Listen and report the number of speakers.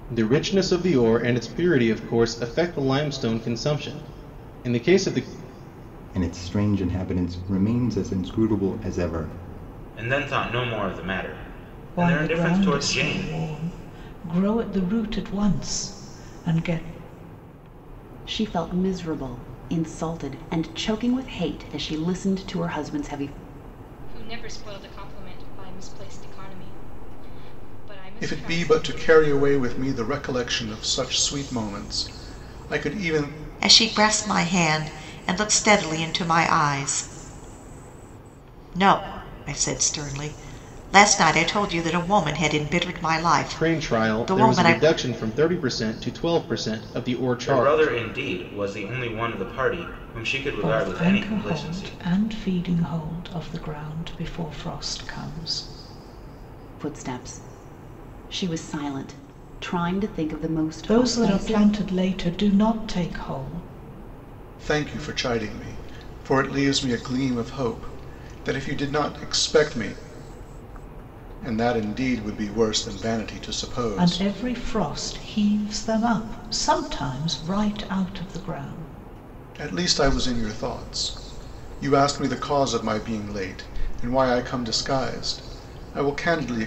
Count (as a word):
eight